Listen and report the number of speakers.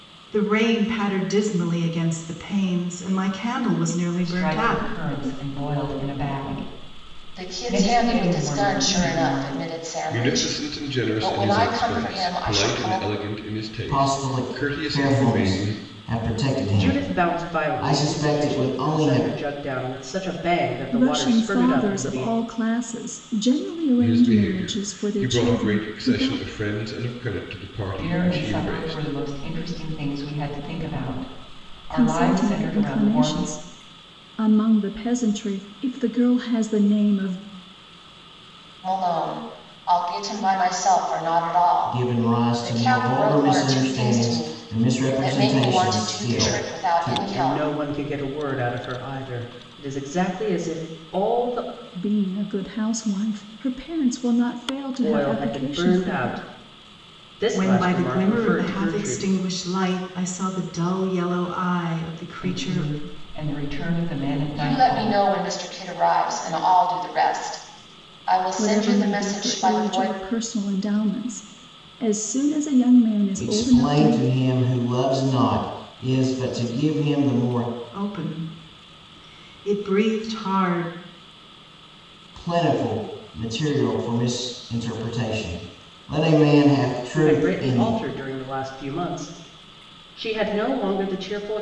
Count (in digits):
7